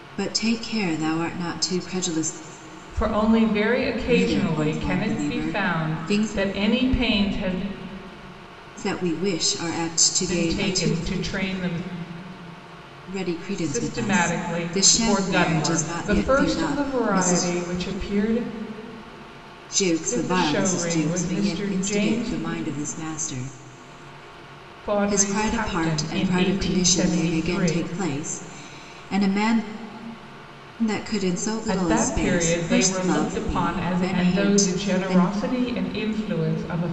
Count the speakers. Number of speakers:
2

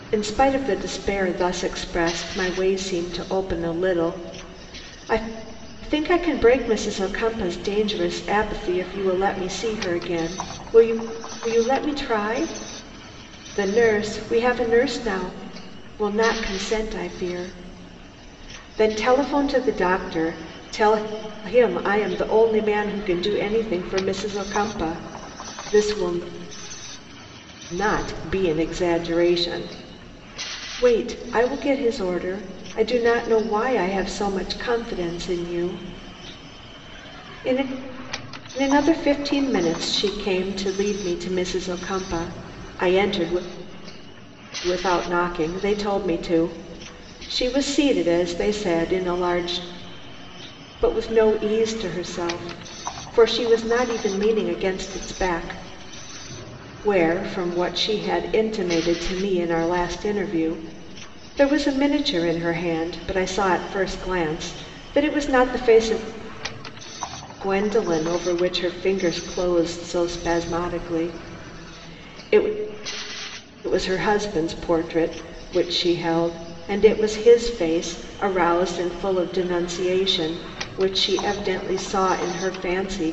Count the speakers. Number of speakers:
1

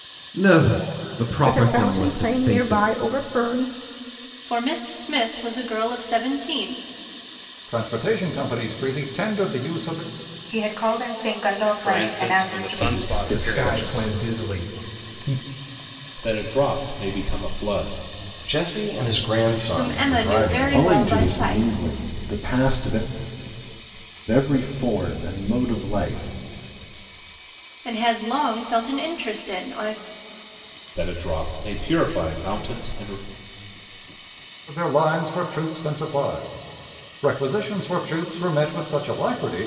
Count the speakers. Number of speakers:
10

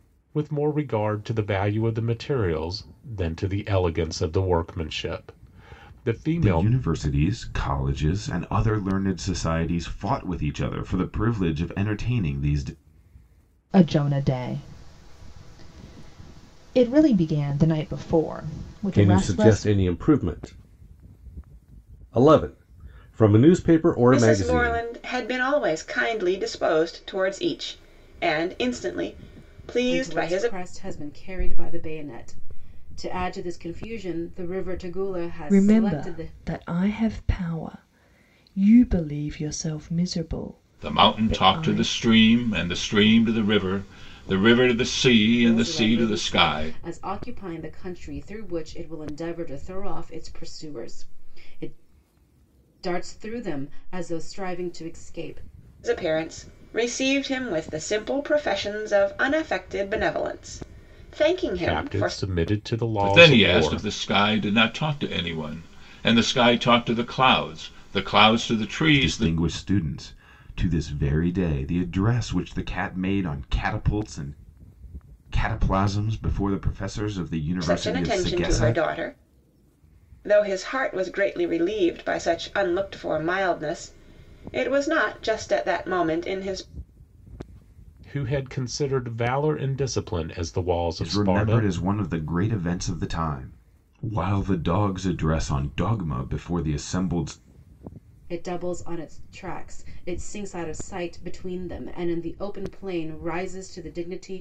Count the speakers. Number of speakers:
8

